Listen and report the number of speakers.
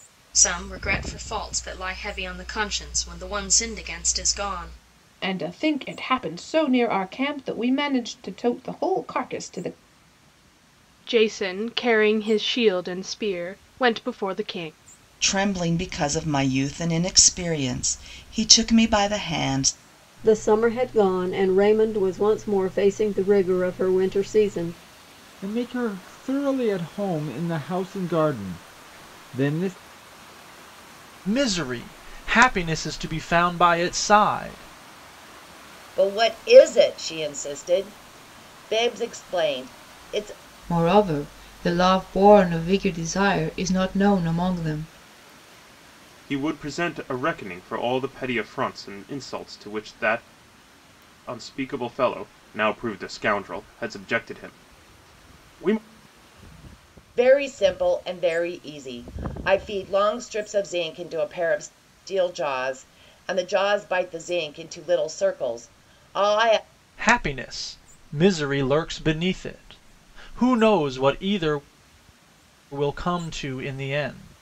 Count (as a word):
ten